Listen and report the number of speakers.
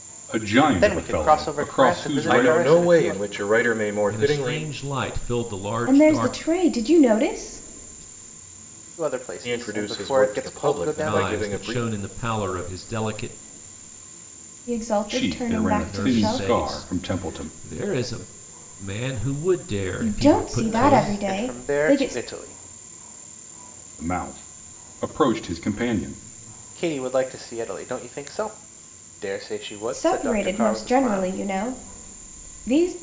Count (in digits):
5